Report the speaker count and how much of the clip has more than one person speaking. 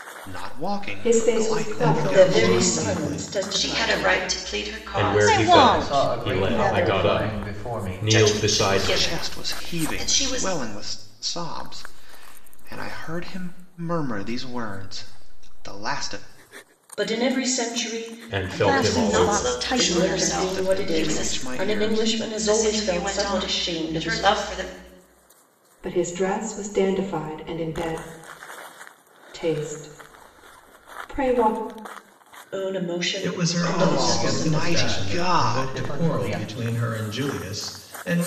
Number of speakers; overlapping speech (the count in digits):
8, about 46%